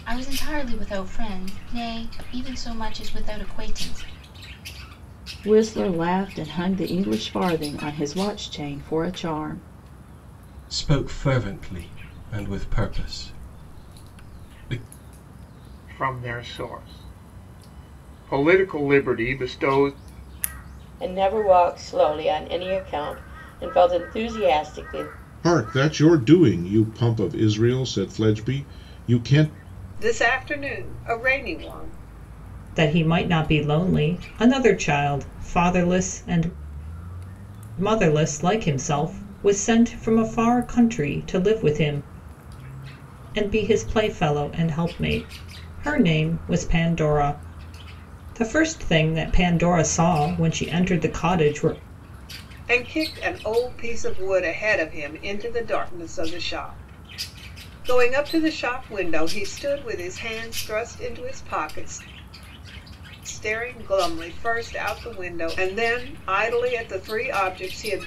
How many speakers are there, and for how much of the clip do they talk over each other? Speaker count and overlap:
eight, no overlap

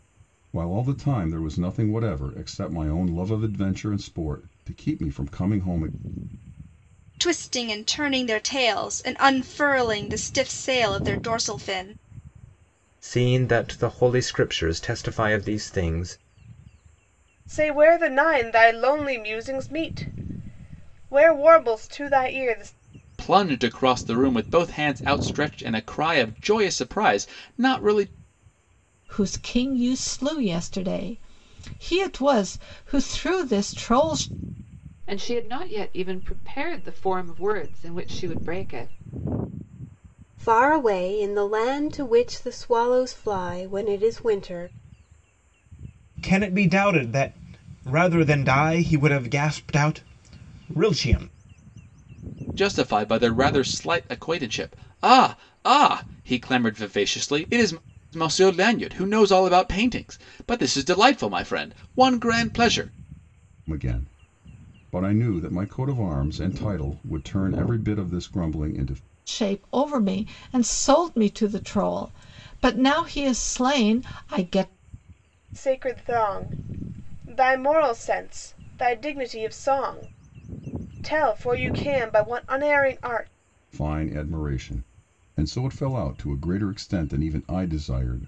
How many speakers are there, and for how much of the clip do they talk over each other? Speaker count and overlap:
nine, no overlap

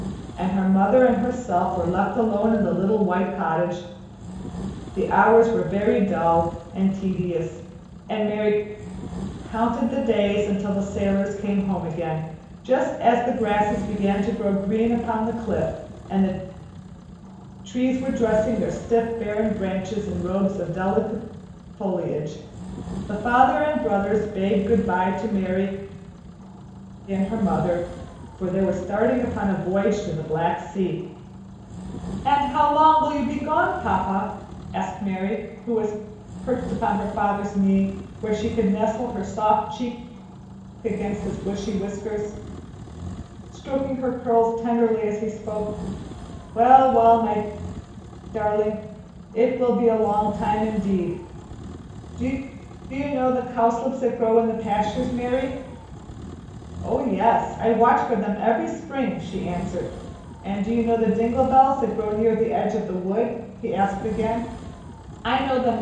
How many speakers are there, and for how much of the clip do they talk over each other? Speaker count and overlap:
one, no overlap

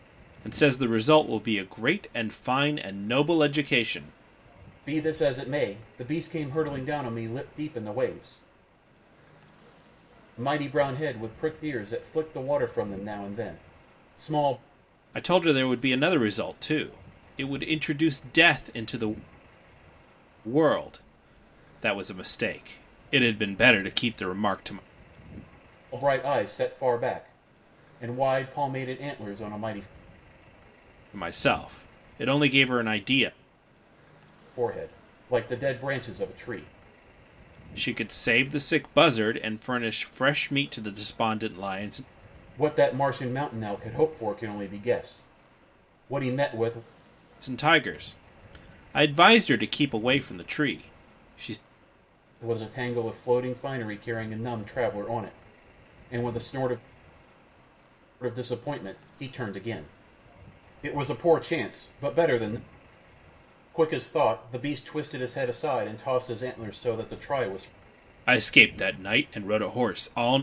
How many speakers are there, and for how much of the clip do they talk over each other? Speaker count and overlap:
two, no overlap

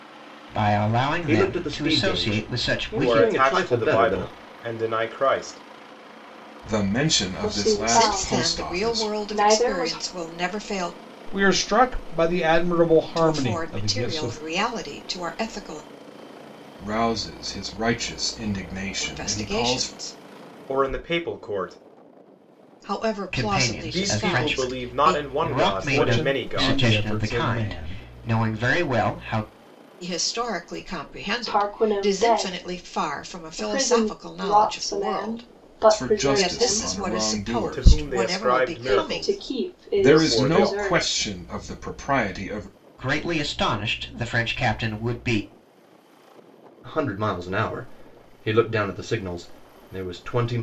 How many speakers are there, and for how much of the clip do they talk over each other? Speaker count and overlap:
seven, about 43%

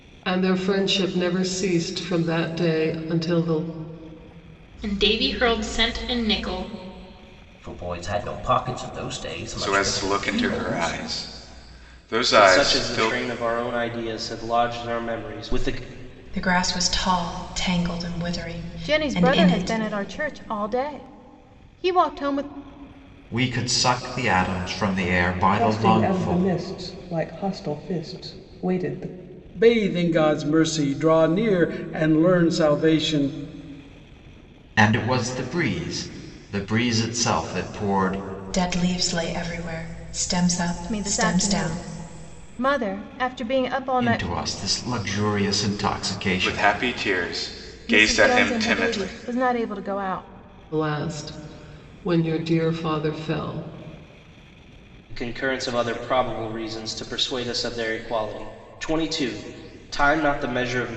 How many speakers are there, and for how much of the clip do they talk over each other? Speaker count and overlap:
ten, about 12%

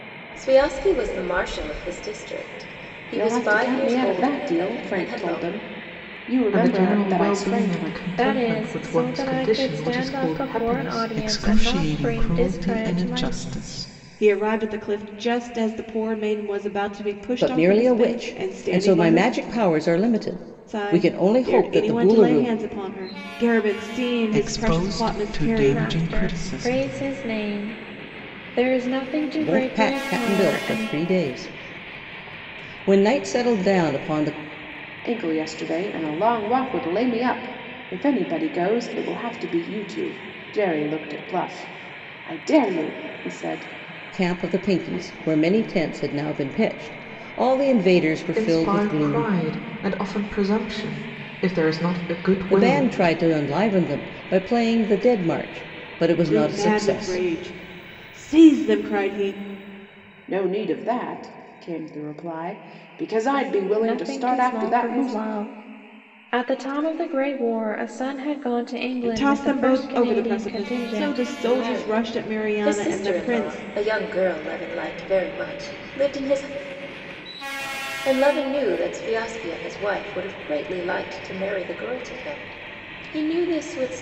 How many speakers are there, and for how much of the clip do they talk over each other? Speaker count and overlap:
seven, about 31%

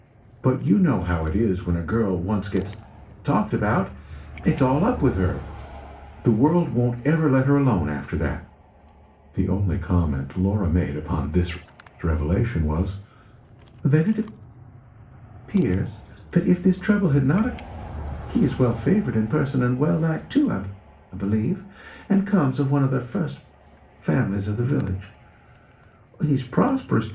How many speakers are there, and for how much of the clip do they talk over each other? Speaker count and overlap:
one, no overlap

